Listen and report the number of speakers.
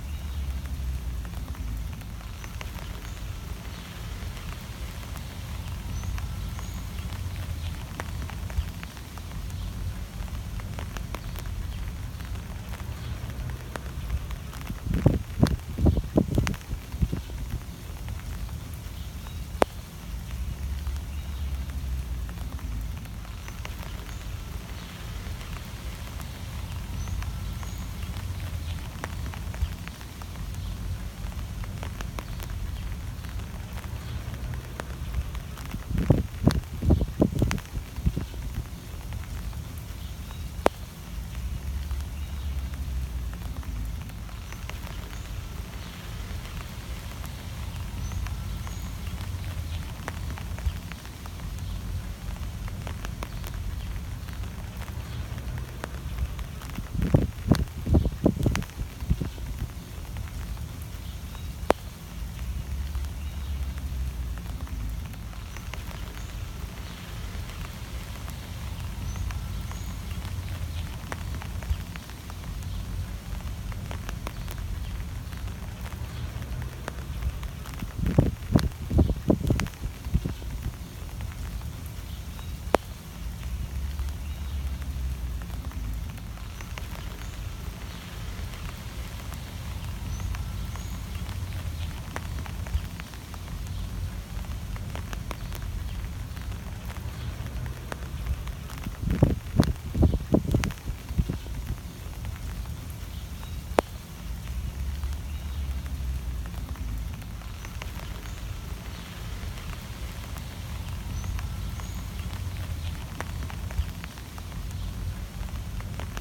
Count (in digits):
0